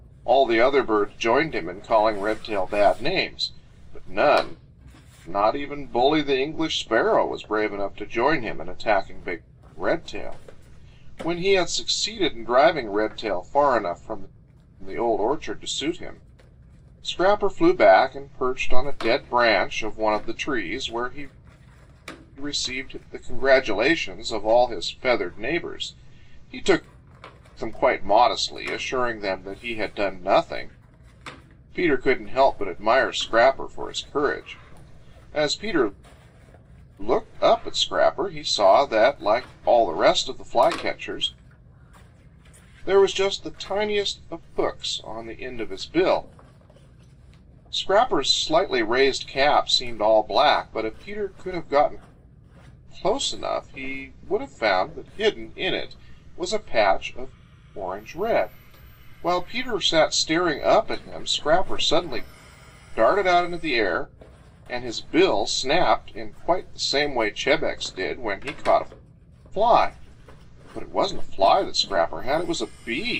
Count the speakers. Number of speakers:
one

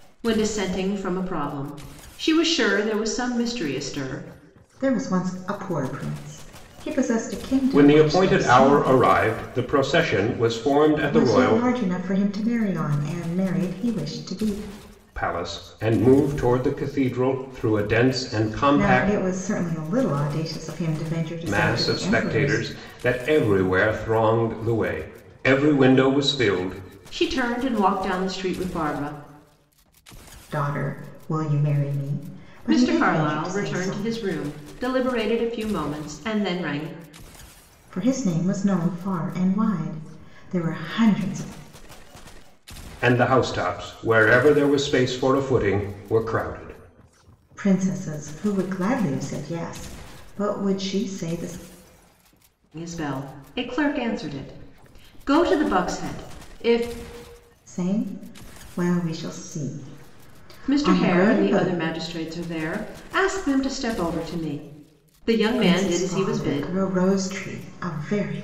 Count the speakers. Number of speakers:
three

